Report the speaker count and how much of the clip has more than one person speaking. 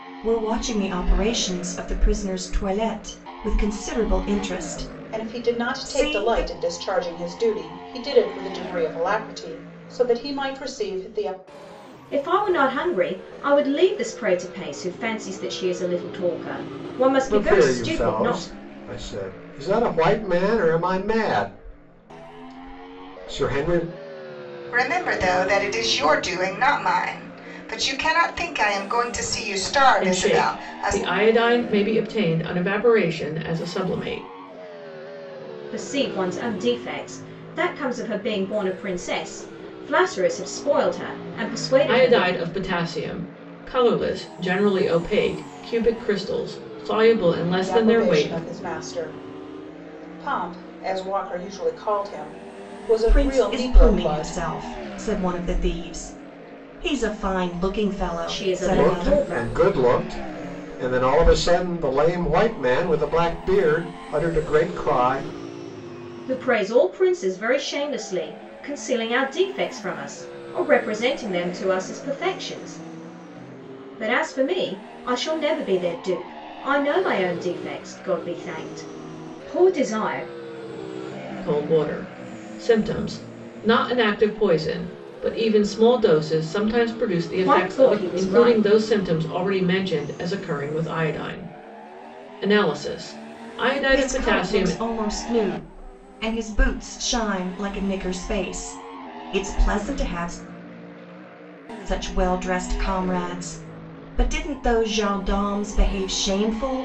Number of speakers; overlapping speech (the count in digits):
6, about 9%